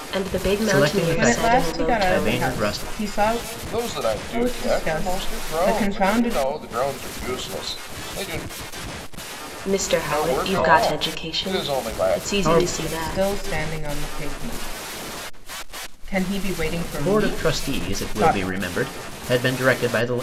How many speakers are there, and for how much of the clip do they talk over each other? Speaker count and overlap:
4, about 45%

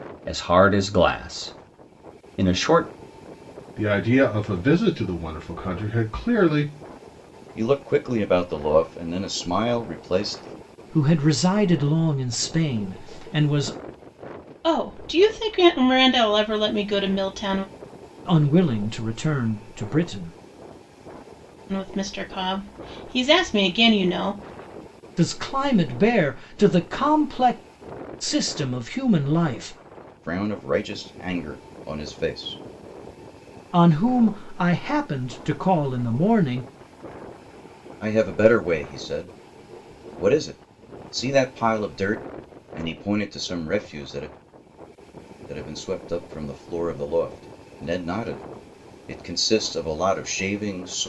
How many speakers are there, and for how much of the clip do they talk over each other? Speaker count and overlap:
5, no overlap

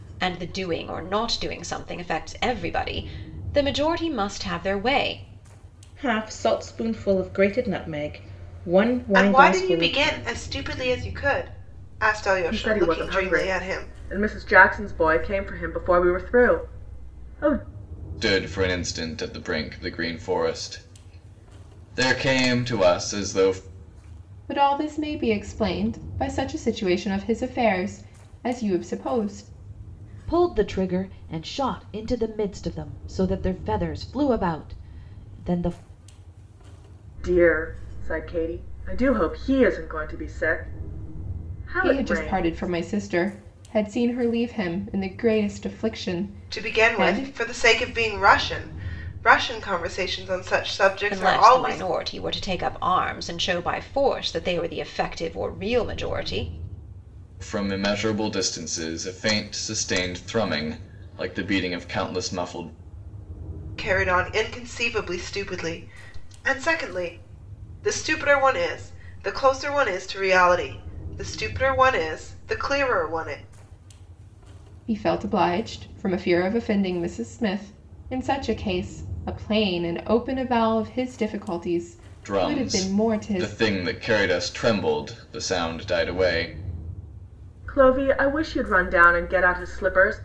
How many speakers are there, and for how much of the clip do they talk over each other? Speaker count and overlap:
7, about 8%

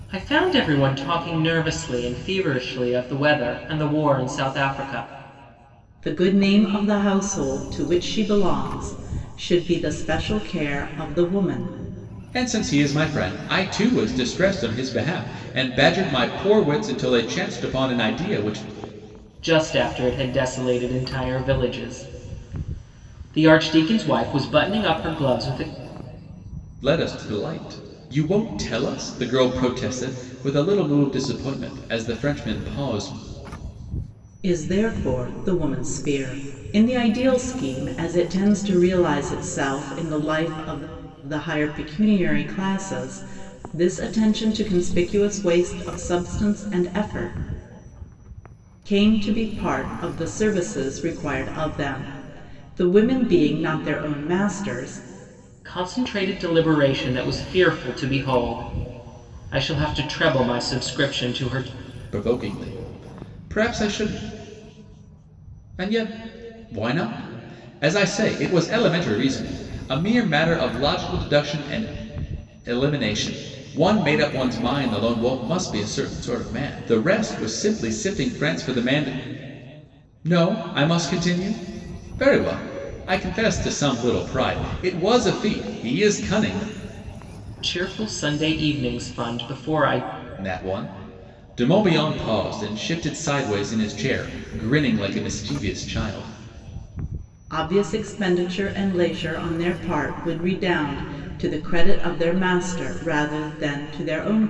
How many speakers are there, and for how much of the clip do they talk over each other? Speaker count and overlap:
3, no overlap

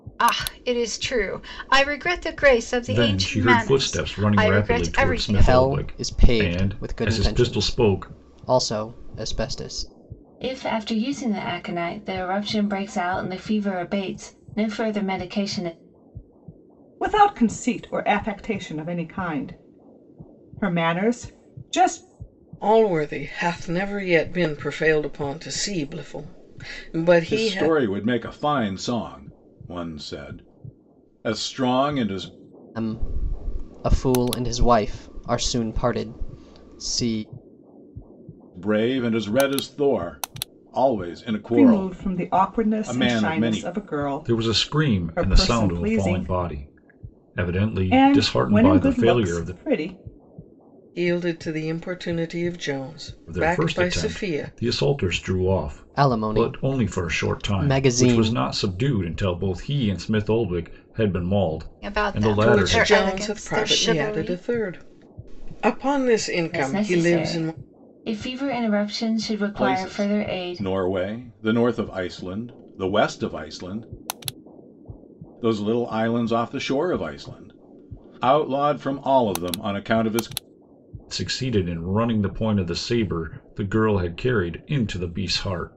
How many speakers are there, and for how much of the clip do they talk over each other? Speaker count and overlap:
7, about 24%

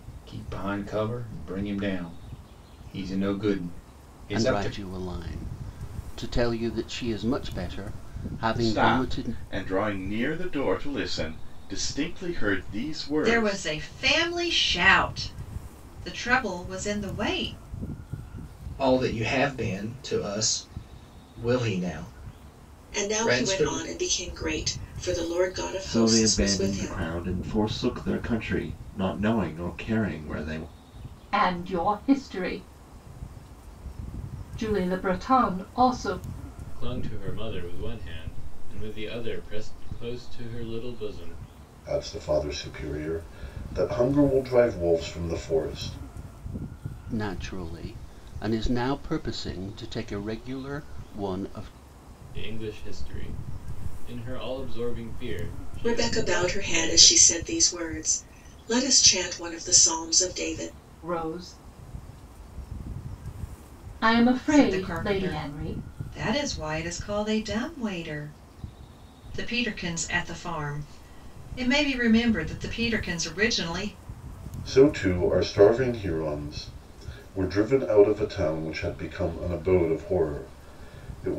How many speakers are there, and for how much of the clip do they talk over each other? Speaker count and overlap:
10, about 8%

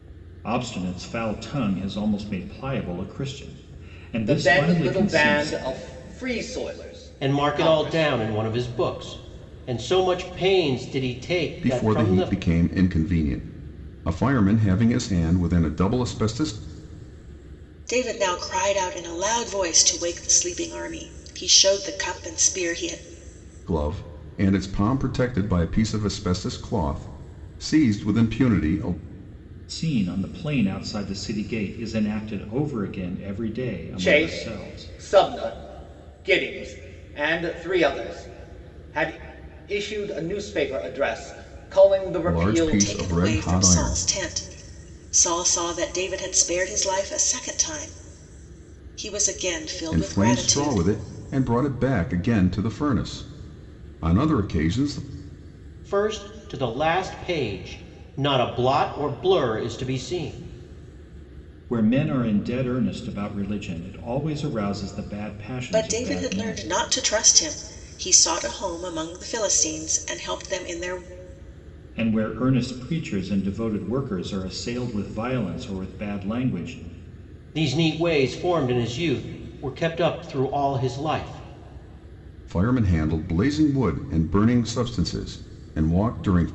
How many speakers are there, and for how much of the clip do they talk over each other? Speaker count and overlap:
5, about 9%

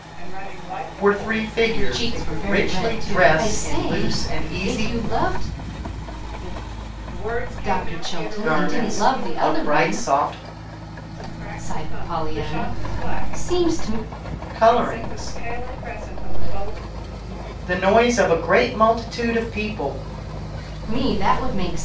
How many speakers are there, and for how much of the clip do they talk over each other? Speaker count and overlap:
3, about 43%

